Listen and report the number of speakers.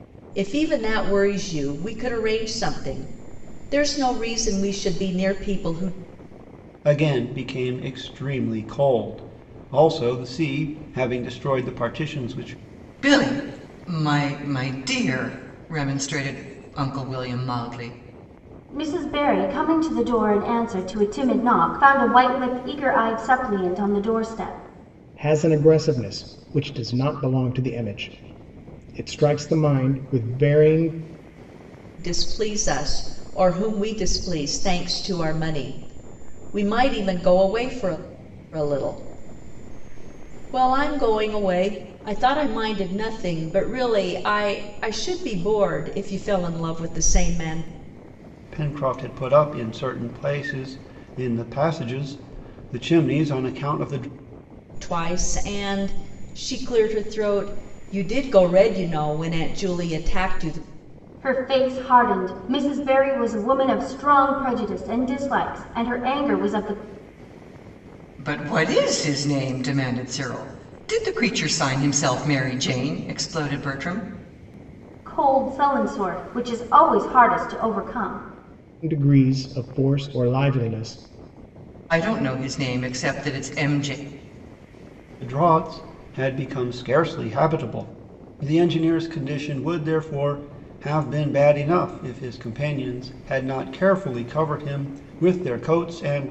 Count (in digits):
5